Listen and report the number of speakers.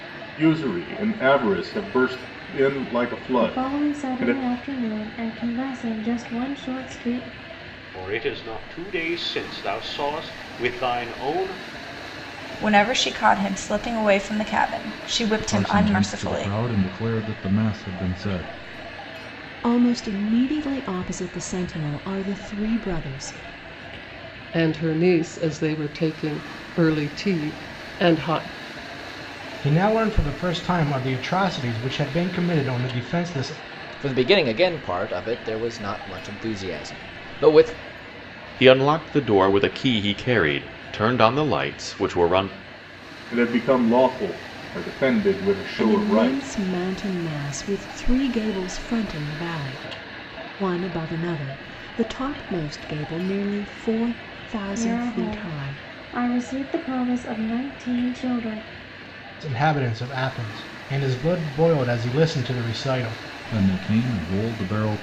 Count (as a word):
ten